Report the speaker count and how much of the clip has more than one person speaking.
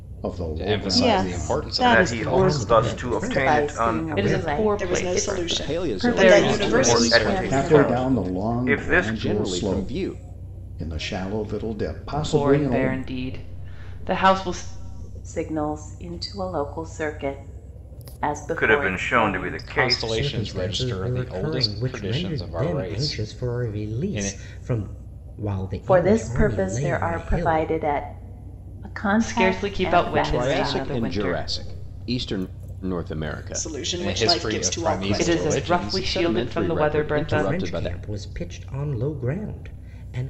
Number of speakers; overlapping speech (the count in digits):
9, about 61%